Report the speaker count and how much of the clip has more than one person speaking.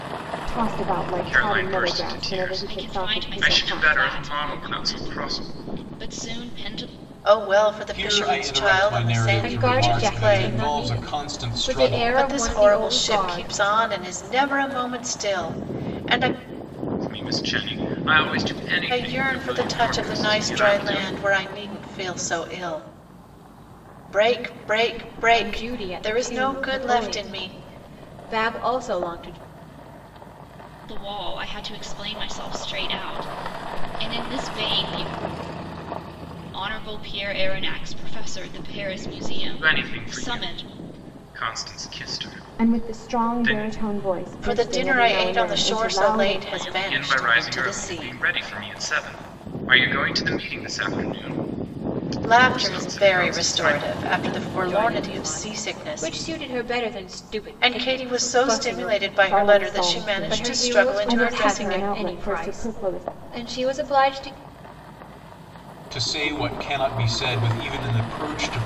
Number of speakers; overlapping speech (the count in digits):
6, about 42%